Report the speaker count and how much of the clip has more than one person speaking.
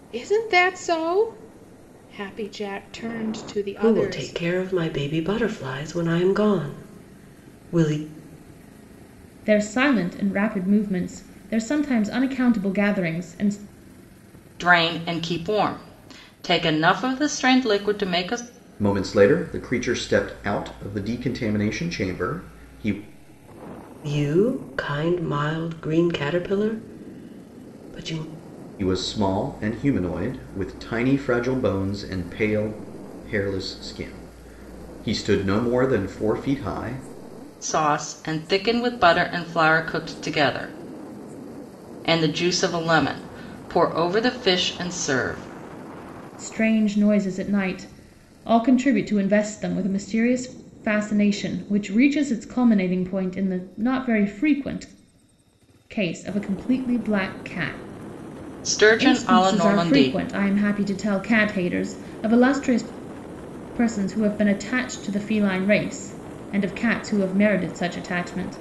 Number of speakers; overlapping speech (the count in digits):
5, about 3%